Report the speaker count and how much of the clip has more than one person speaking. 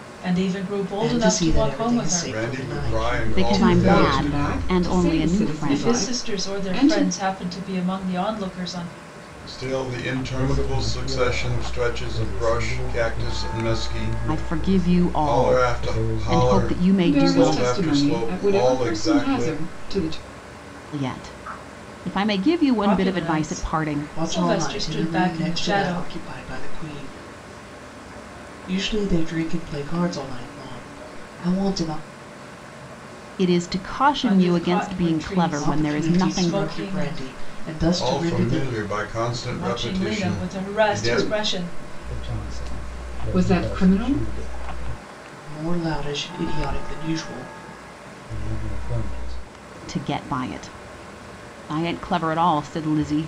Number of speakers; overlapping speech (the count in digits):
6, about 50%